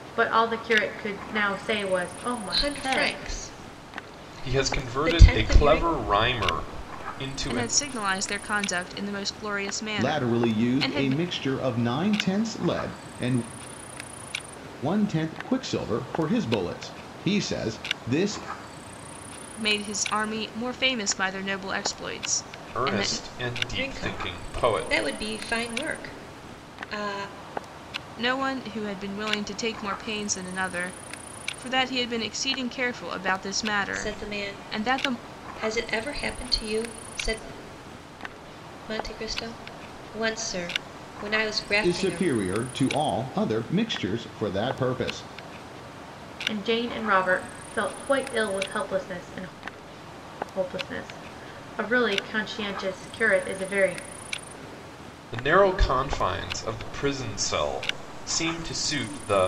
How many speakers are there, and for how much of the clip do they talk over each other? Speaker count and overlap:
five, about 12%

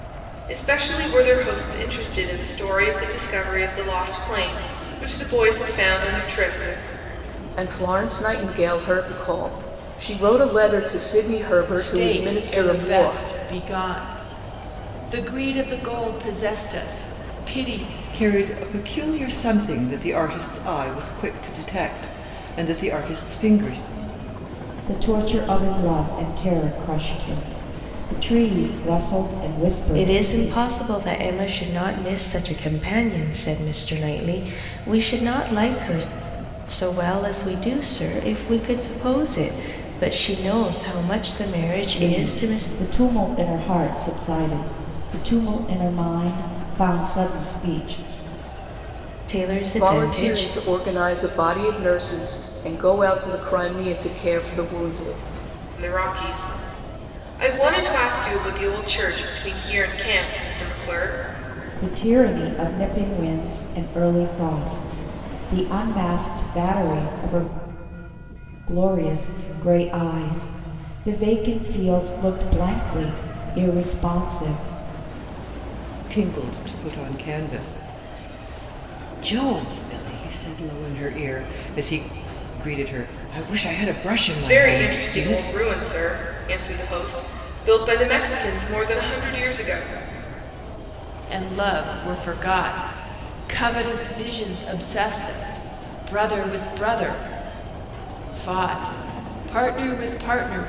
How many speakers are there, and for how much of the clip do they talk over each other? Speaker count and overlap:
six, about 5%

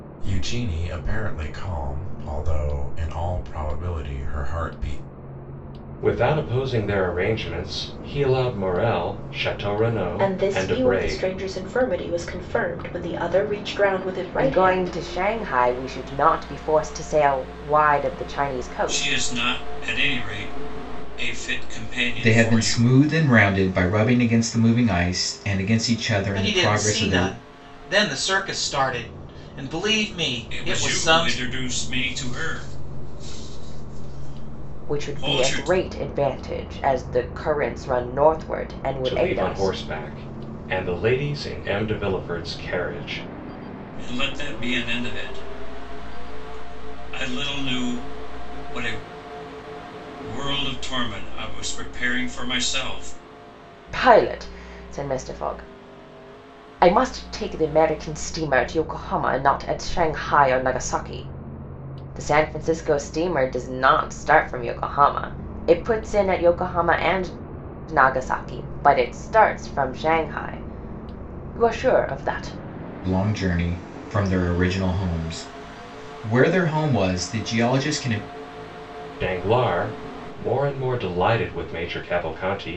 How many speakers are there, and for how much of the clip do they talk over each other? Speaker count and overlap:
seven, about 8%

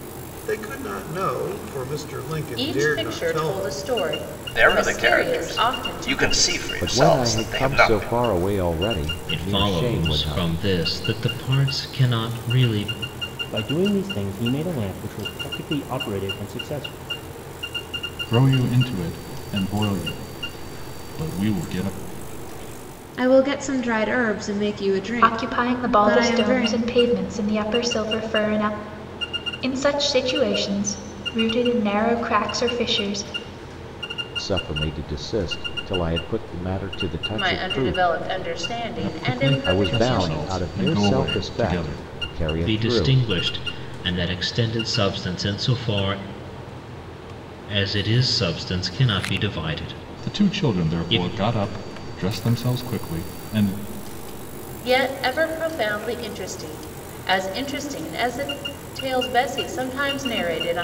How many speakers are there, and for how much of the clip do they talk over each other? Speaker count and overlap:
nine, about 21%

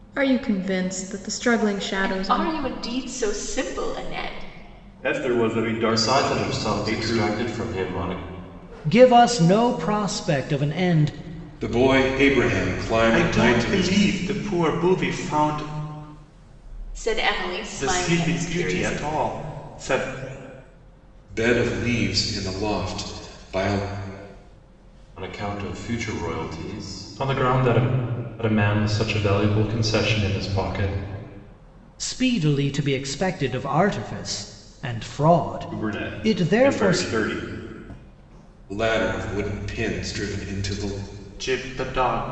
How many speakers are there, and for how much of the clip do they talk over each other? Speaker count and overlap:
seven, about 13%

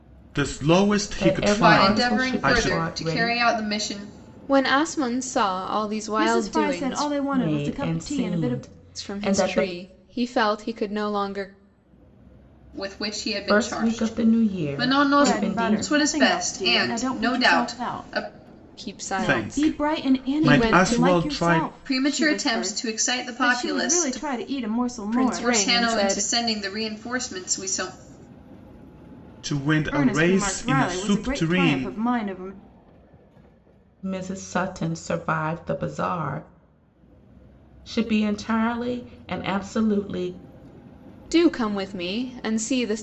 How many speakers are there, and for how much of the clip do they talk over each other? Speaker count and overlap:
five, about 43%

